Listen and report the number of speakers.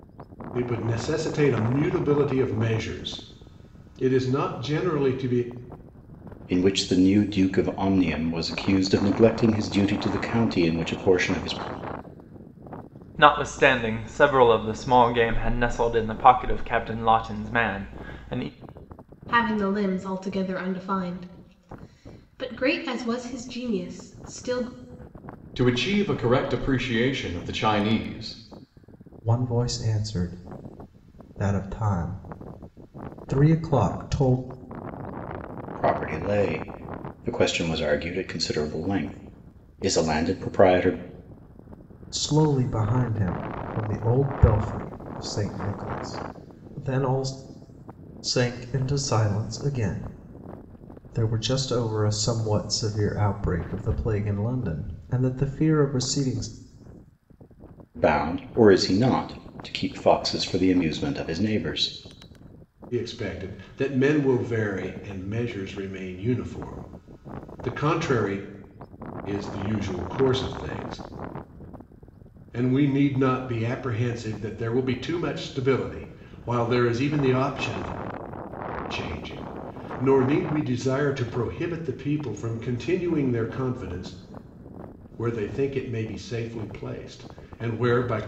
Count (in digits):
6